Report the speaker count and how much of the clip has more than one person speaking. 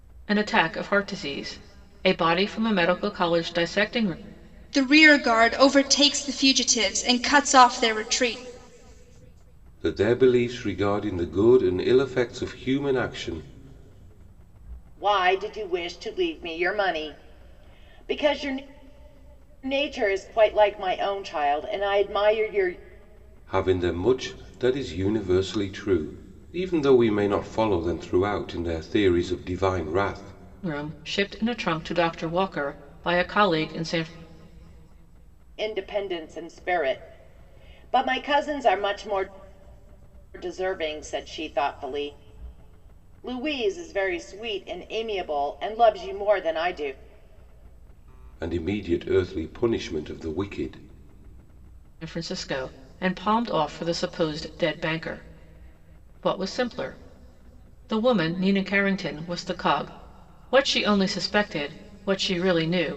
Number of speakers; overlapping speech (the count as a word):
four, no overlap